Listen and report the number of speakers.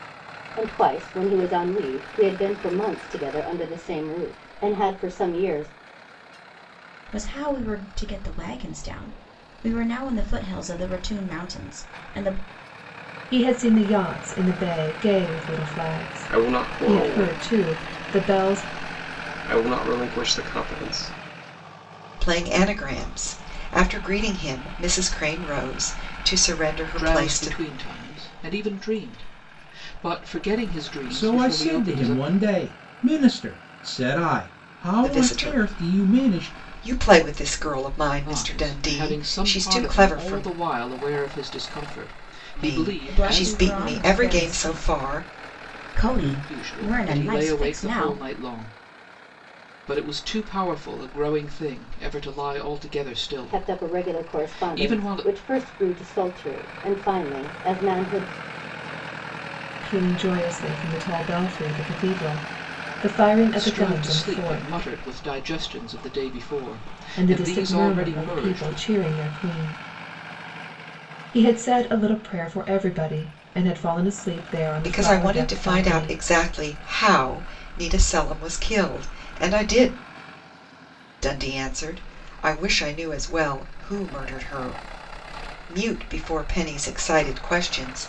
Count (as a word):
seven